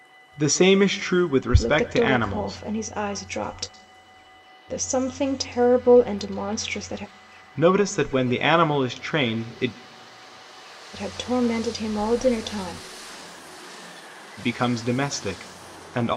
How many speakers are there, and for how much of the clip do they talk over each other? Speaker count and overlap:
2, about 7%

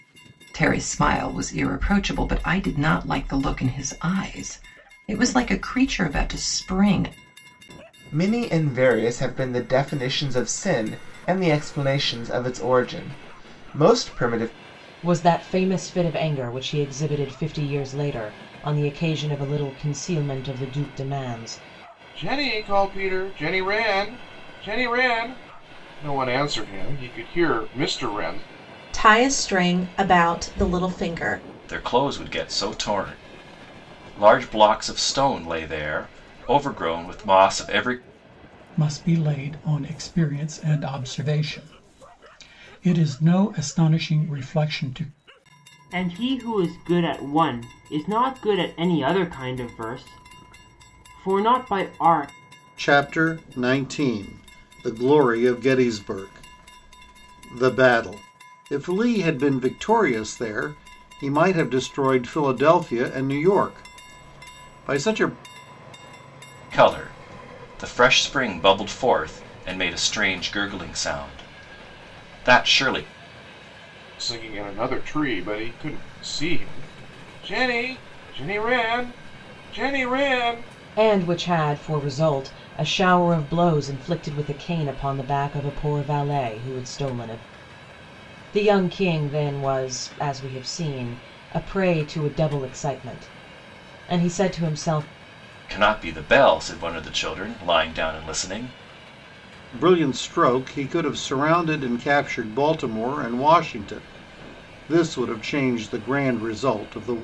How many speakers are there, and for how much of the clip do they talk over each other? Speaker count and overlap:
9, no overlap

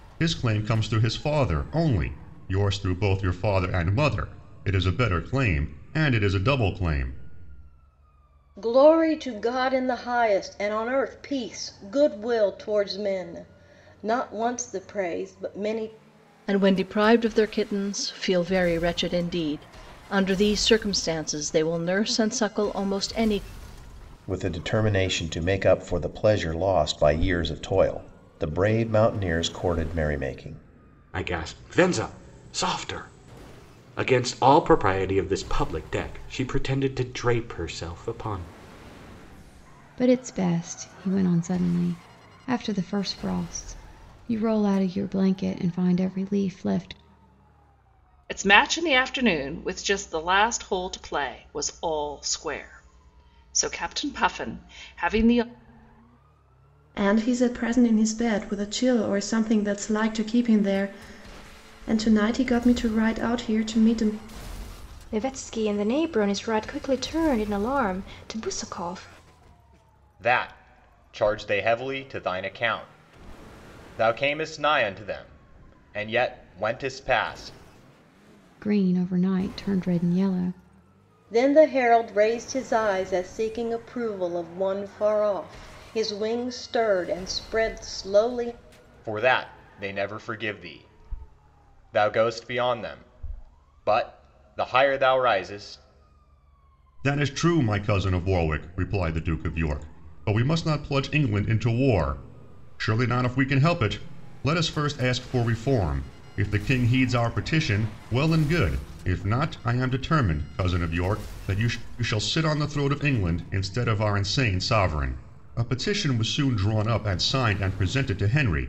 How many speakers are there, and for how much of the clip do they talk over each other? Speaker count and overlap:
10, no overlap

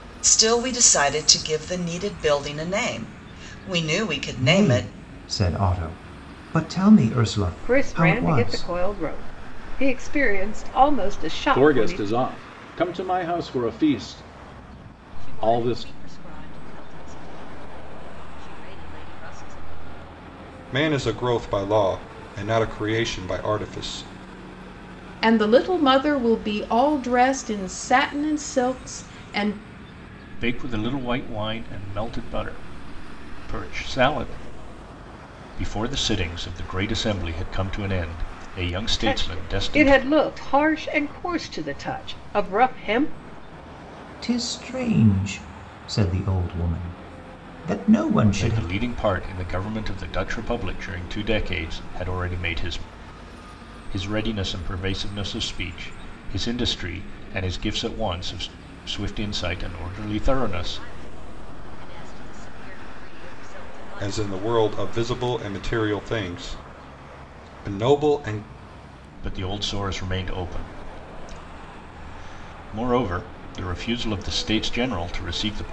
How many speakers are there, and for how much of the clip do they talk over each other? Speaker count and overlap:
8, about 8%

